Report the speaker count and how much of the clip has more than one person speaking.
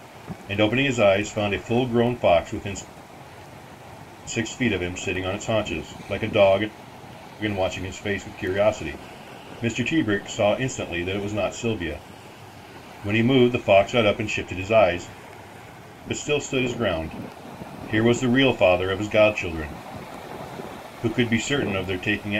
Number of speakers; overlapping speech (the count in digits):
1, no overlap